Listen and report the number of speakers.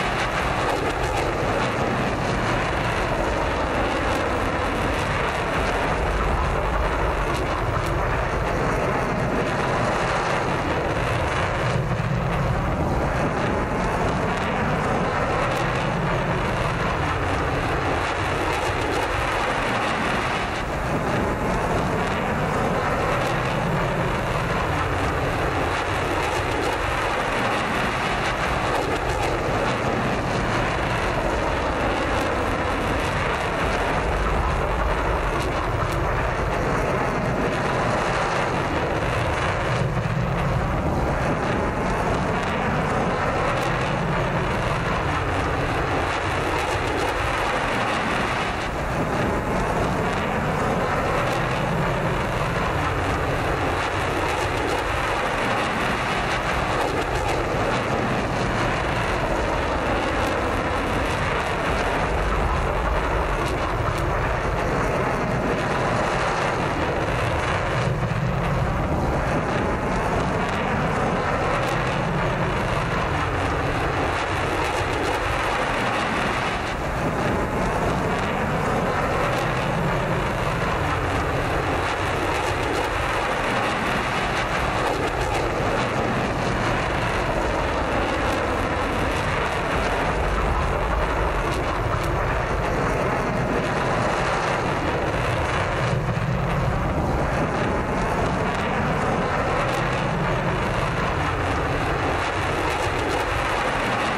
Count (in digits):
0